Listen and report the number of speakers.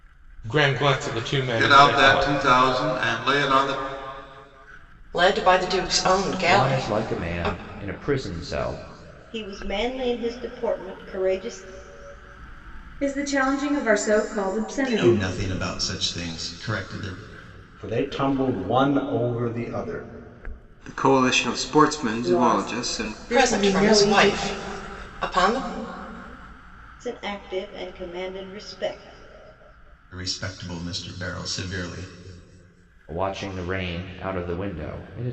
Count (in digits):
9